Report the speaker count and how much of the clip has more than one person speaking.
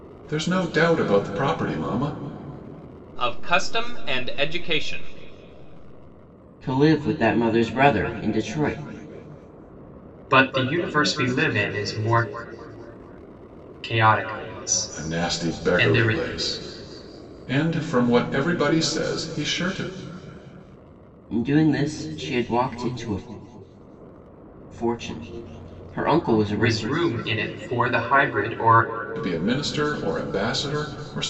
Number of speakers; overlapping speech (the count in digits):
4, about 5%